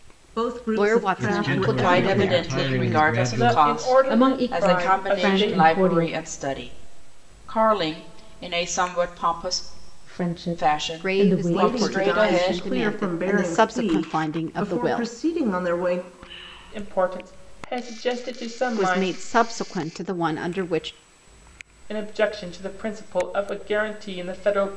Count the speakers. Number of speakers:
six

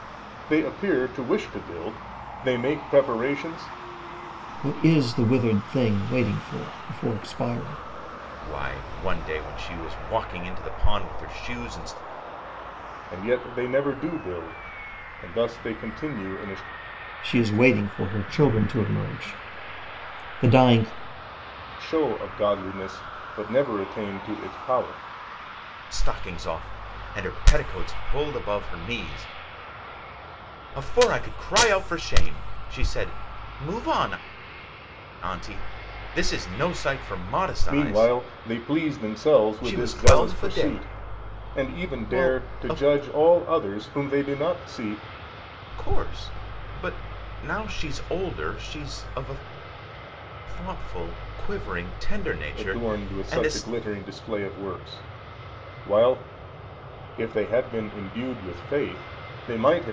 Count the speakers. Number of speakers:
three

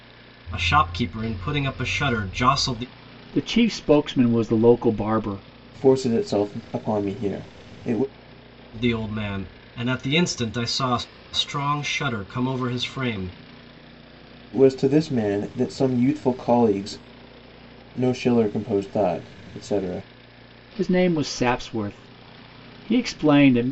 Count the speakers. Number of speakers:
three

